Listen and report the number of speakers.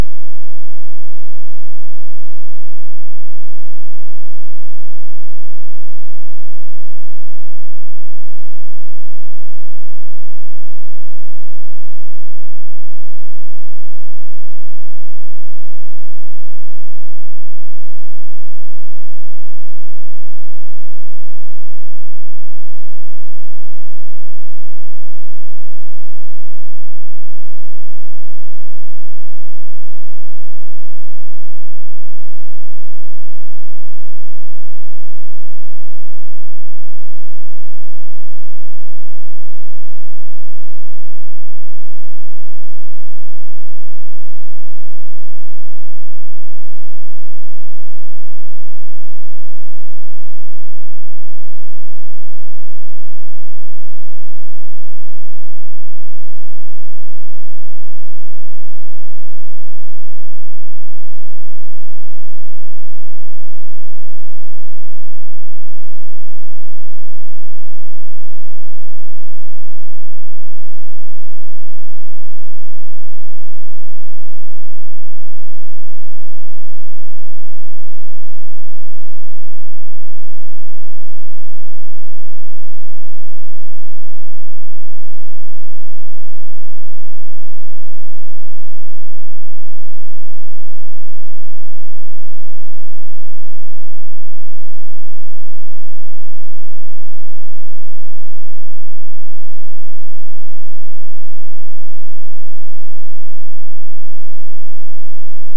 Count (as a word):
zero